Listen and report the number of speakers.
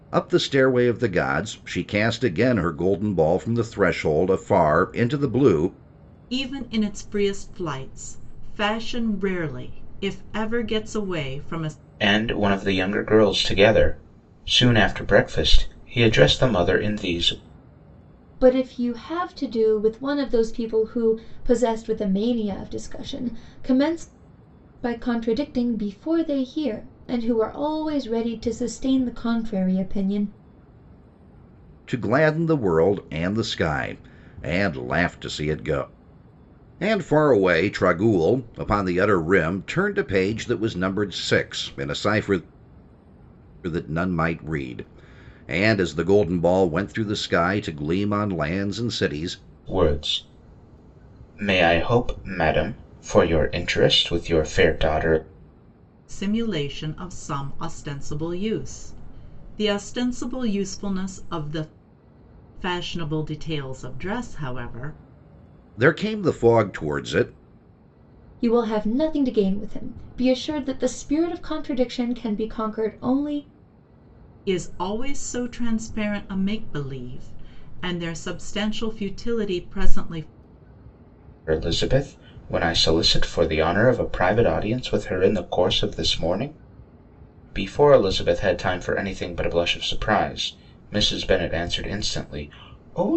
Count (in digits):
4